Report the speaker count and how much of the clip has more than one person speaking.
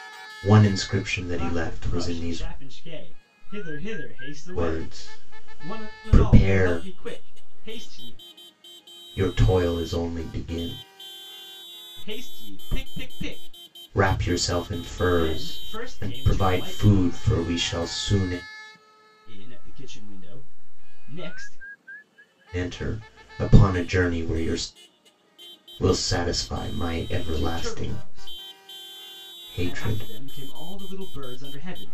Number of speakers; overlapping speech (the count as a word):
two, about 22%